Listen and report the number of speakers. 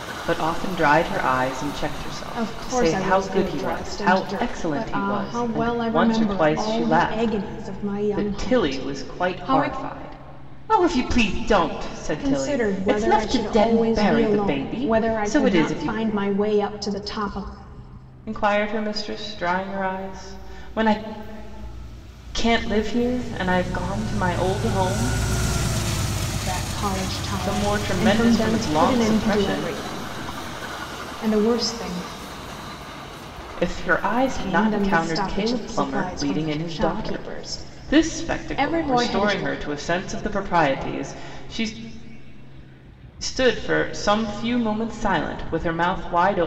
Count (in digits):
2